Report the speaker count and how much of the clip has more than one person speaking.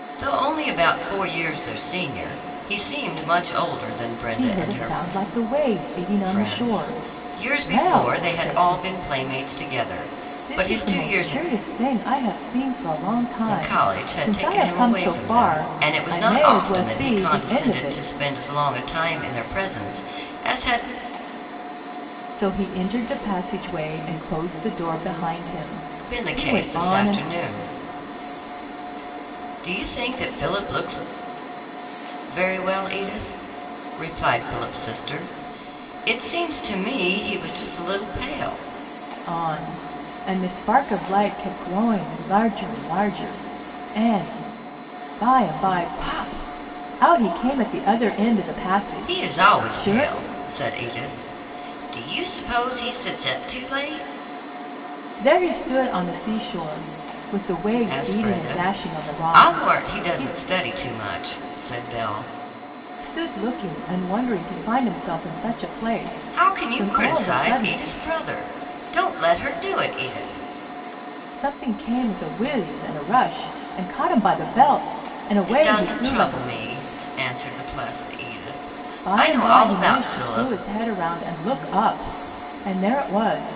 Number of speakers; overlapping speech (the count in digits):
2, about 21%